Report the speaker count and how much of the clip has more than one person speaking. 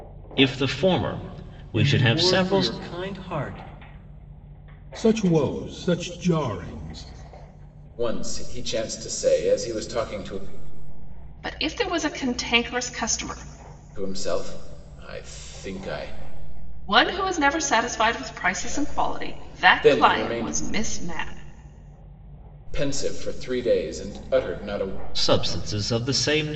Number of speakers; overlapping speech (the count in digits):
5, about 11%